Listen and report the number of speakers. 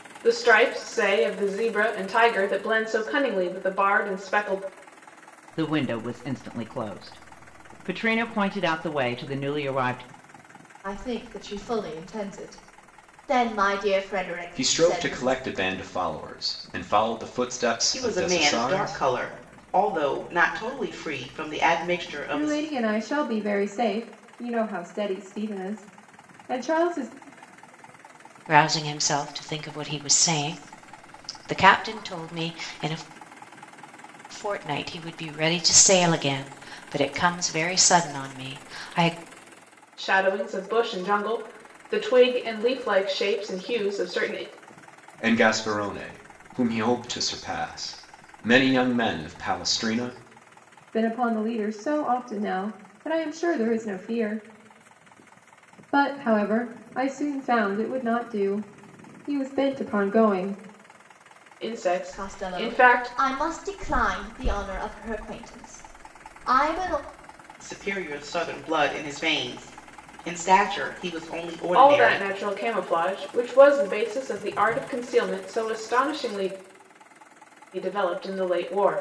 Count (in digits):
7